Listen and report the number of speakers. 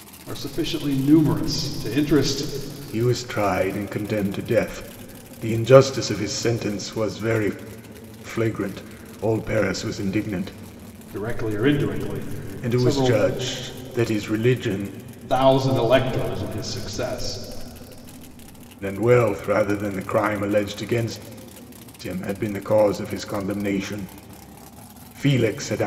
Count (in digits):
2